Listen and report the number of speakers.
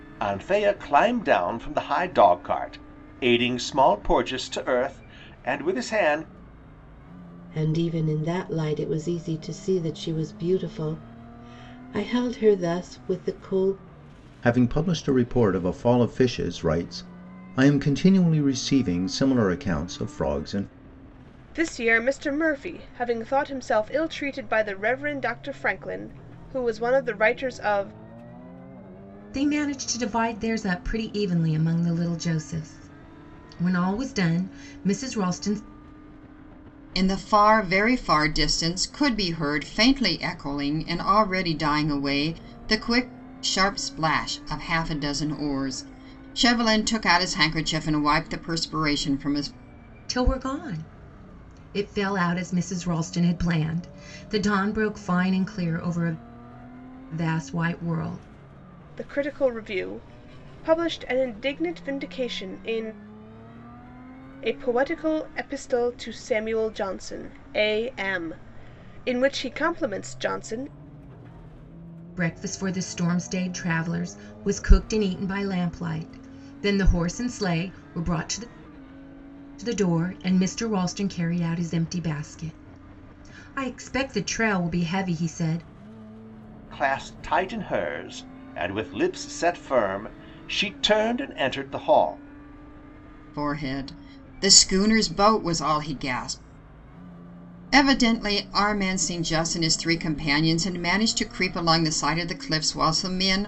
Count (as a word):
six